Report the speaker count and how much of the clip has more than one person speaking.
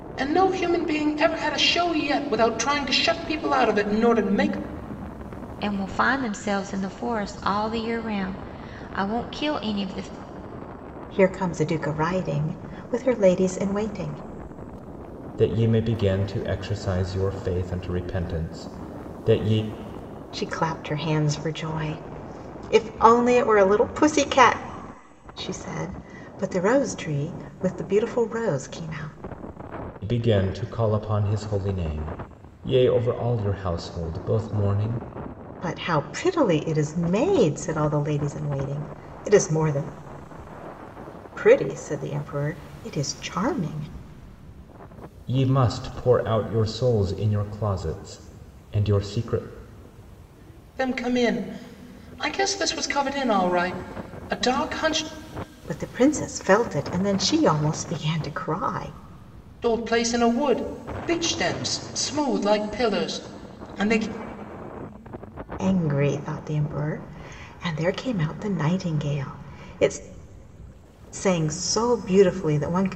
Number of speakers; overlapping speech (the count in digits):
4, no overlap